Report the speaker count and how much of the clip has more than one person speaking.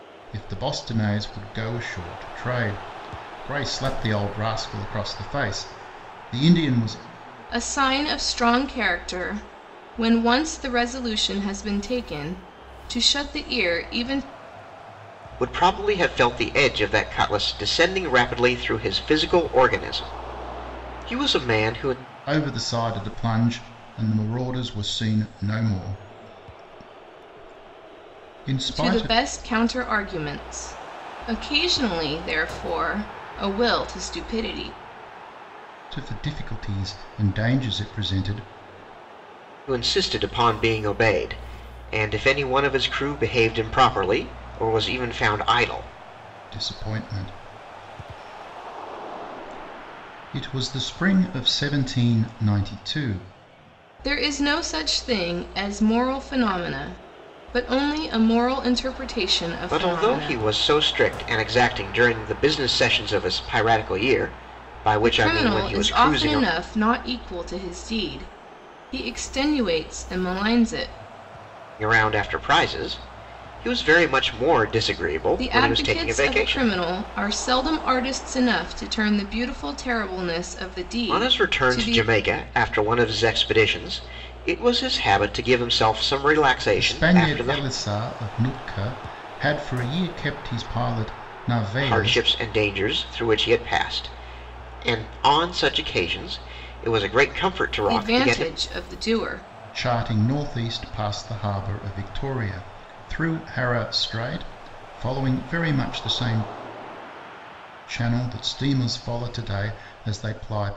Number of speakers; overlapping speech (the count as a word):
three, about 6%